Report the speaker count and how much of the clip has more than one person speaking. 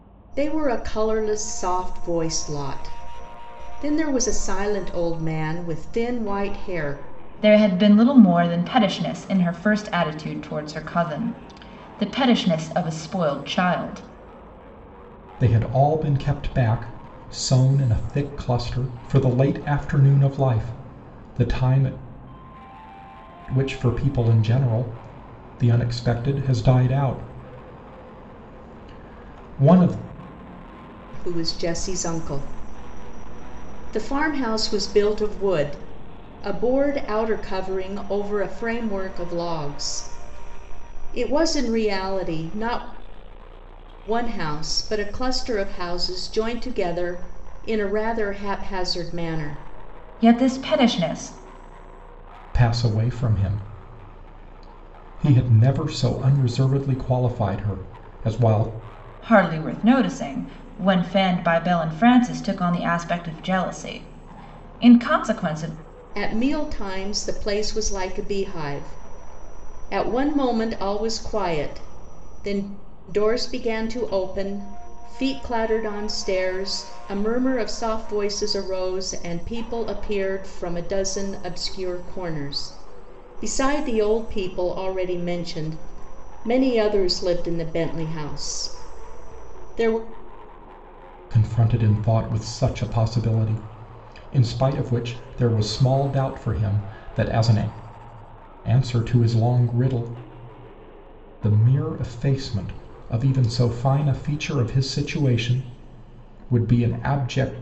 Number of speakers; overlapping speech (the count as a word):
three, no overlap